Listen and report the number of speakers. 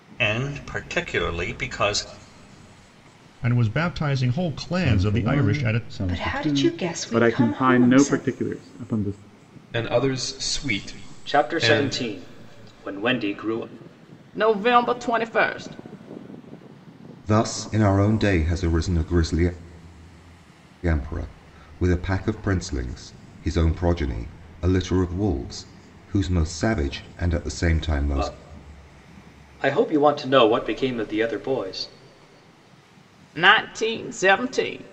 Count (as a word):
nine